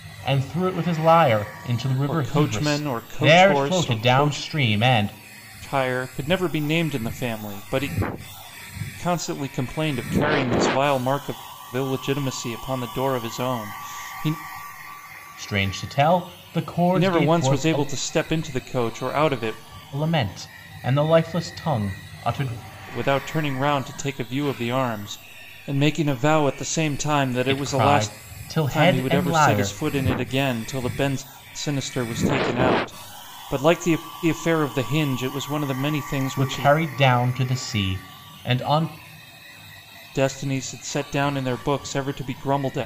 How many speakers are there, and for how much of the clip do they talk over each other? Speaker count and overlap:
two, about 13%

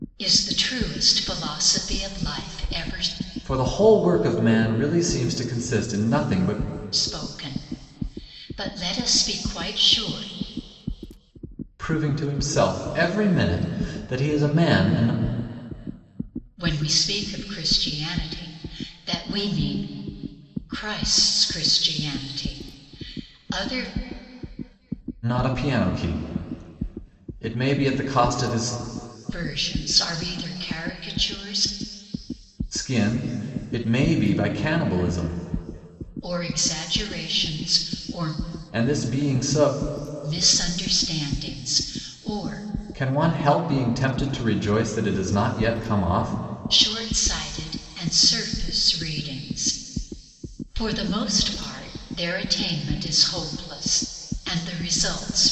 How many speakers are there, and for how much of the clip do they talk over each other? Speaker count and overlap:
two, no overlap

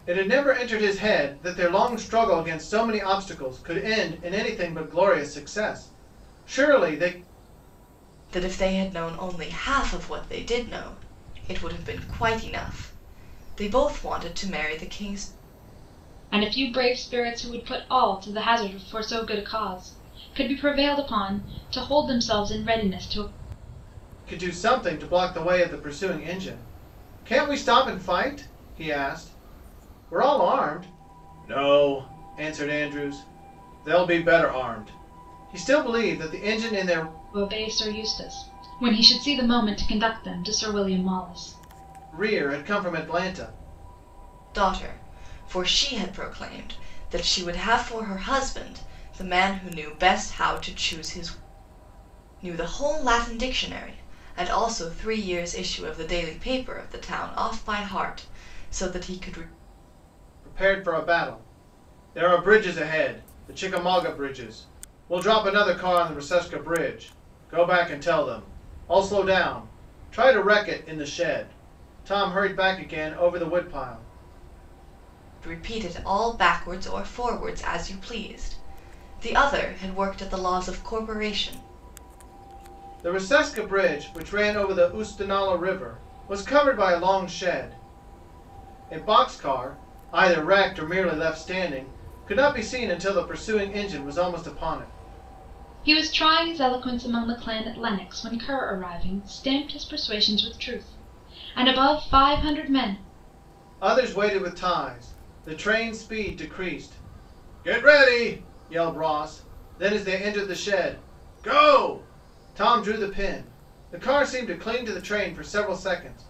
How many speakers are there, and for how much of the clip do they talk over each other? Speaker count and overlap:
three, no overlap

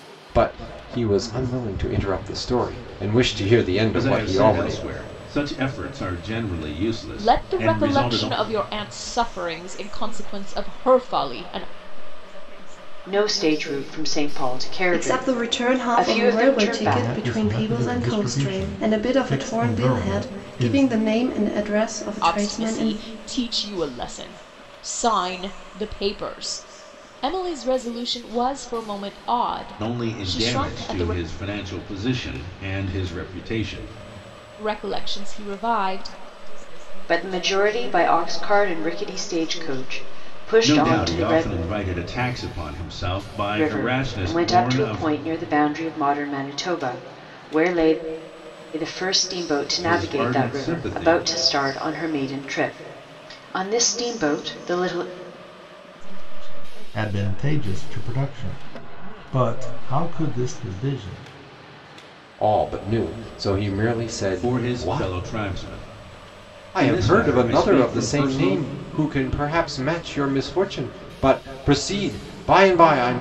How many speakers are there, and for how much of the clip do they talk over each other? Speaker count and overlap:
seven, about 36%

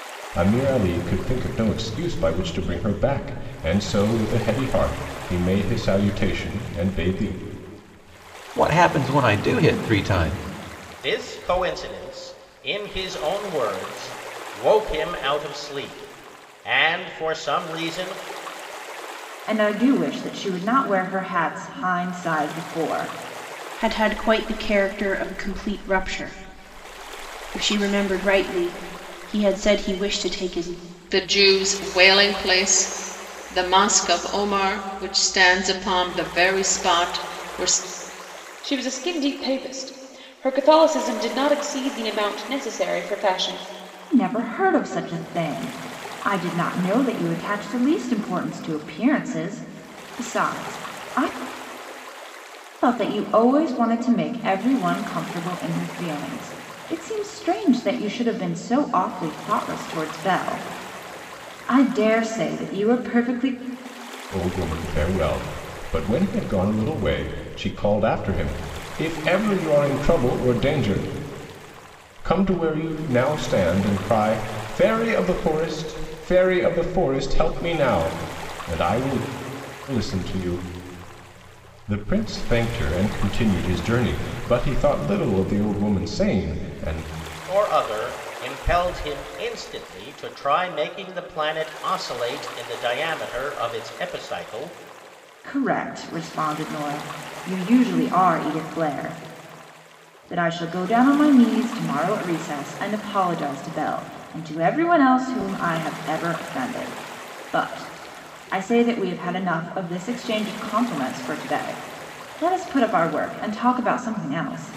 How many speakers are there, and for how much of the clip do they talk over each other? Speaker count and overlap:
seven, no overlap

